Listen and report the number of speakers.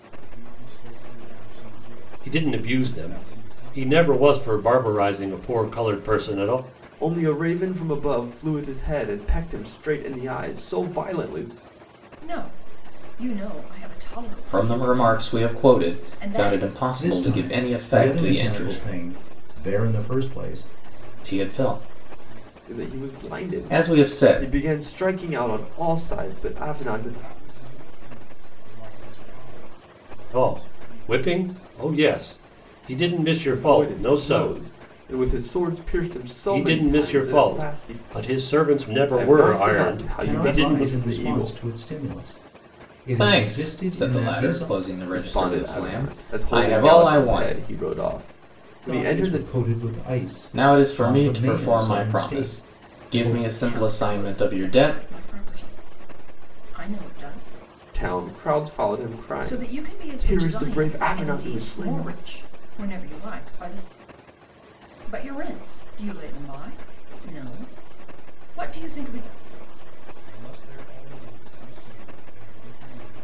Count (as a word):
six